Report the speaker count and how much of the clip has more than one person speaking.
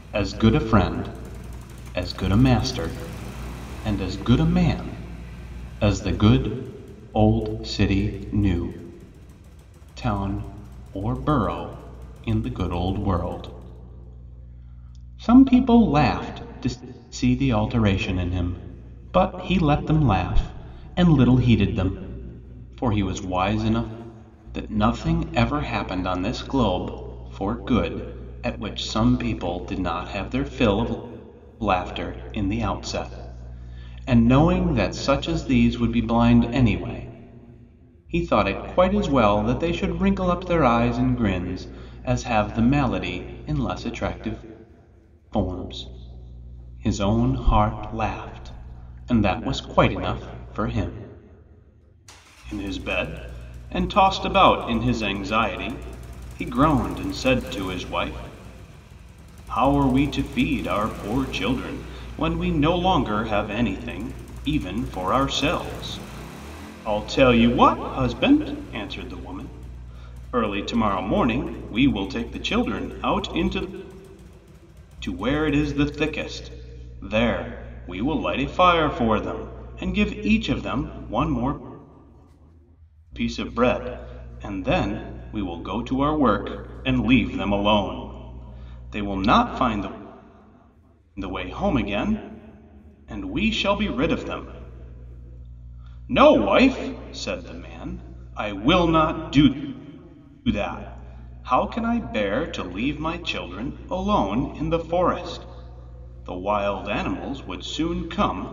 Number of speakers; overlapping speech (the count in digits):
1, no overlap